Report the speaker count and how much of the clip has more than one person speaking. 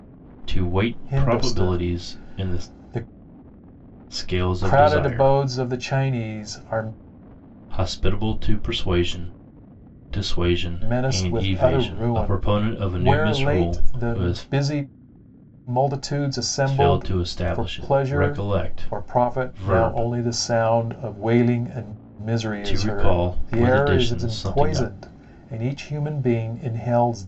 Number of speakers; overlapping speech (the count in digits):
2, about 41%